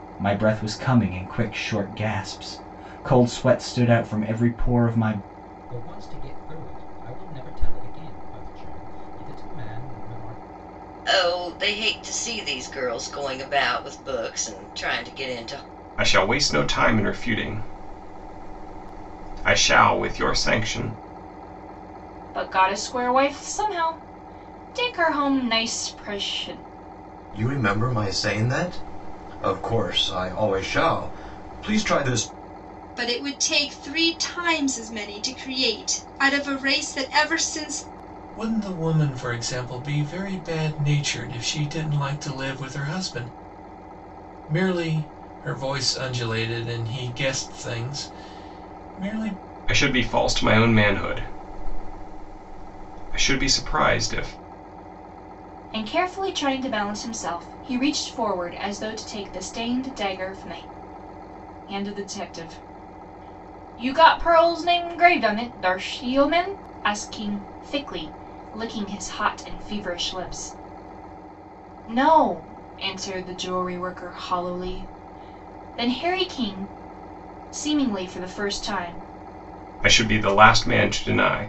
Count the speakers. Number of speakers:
8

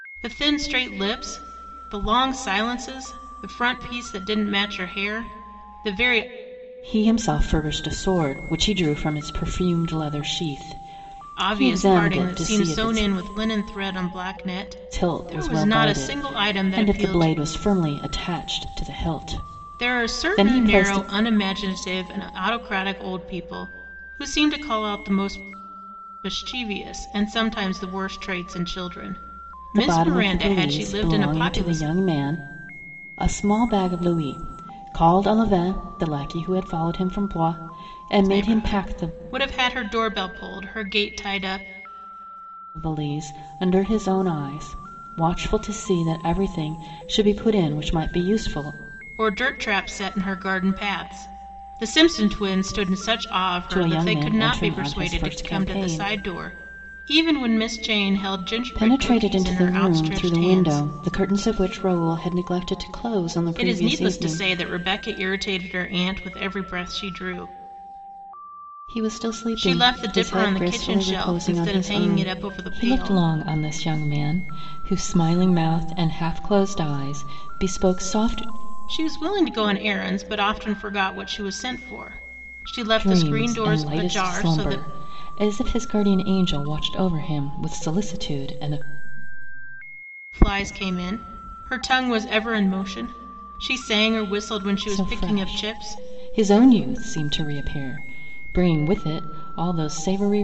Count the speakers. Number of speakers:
2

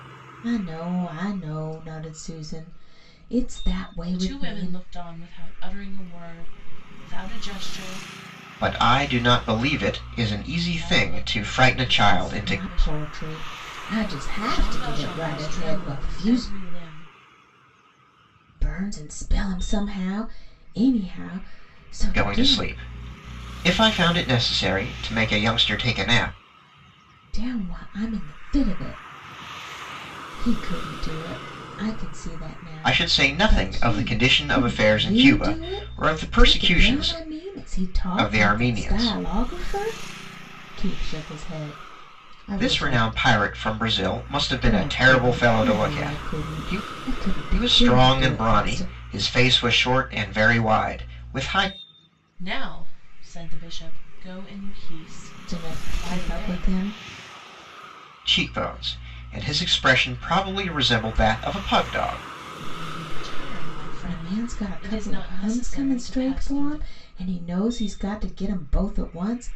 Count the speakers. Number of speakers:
3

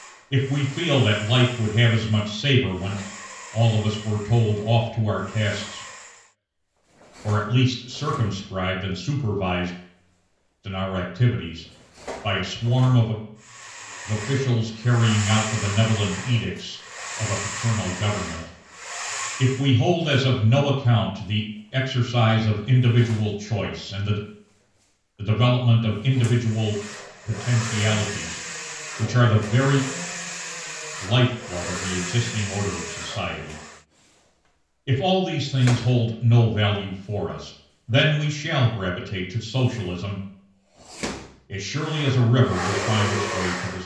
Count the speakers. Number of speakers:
1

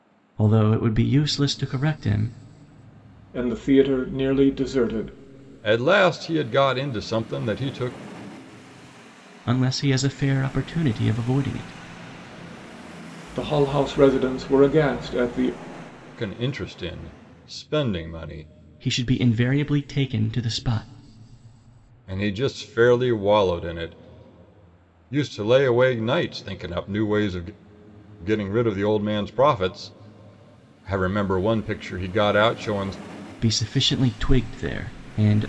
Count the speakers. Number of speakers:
3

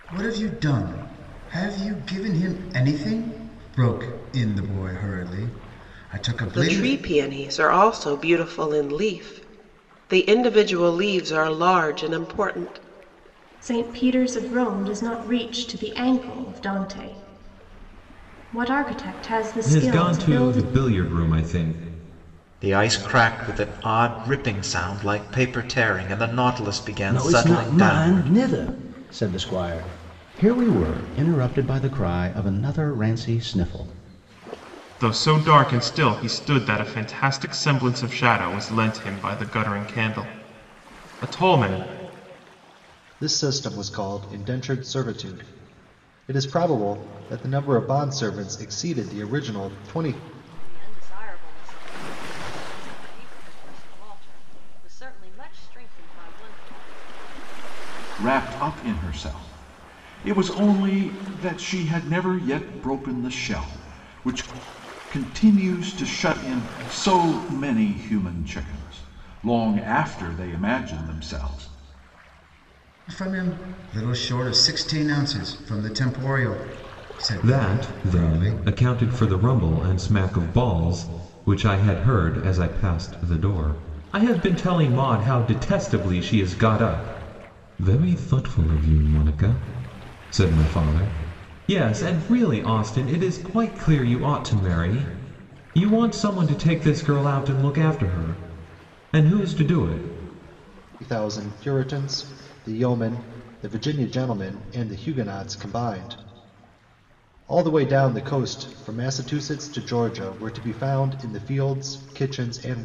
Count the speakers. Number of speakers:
10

